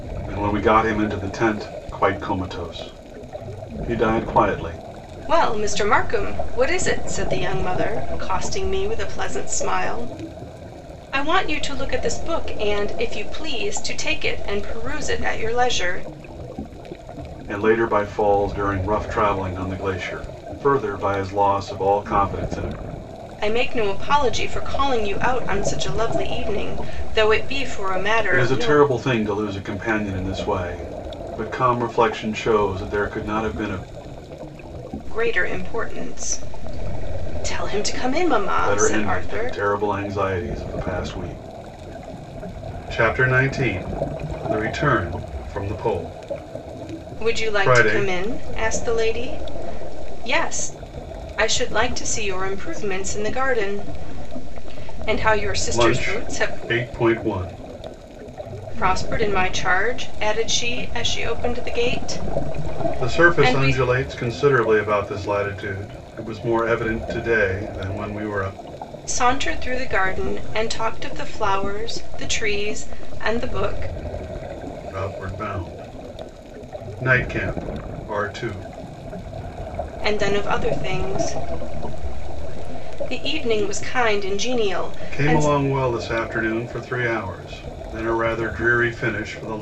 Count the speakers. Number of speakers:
two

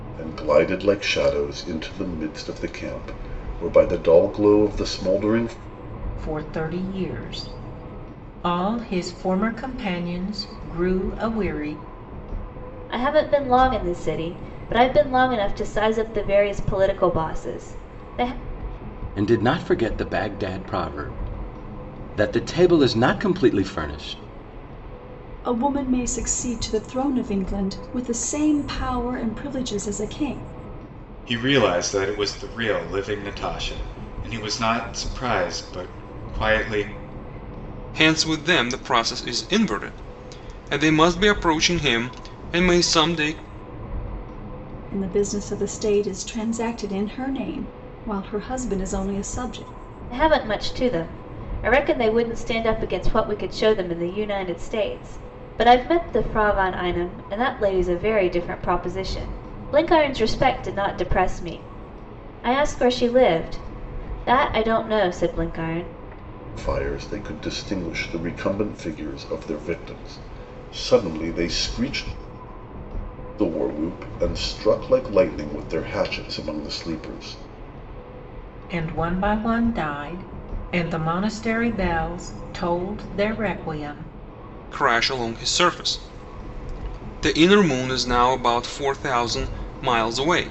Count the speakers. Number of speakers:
seven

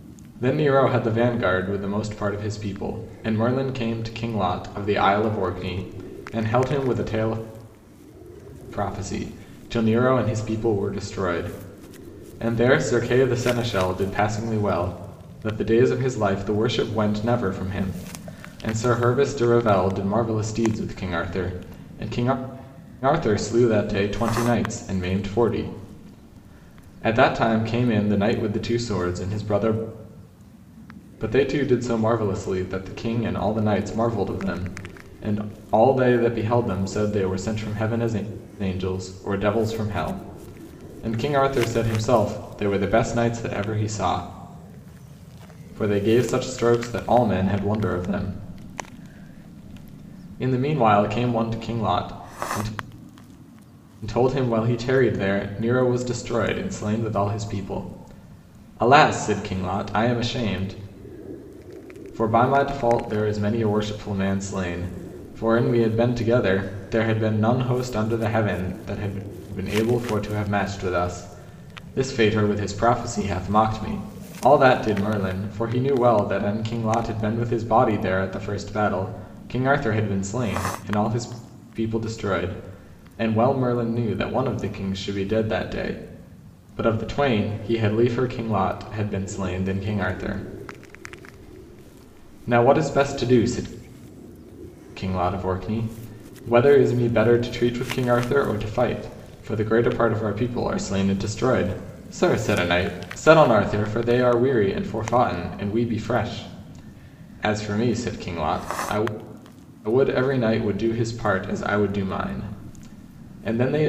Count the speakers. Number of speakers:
one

